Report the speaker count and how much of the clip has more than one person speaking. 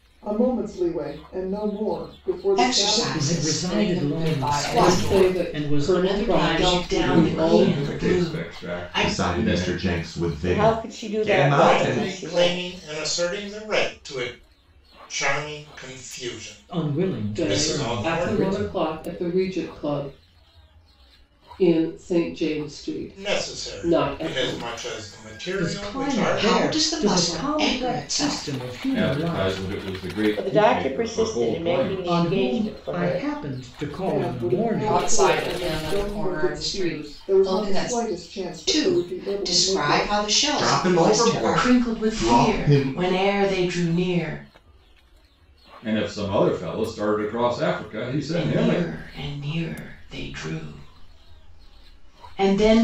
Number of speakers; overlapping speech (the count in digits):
10, about 55%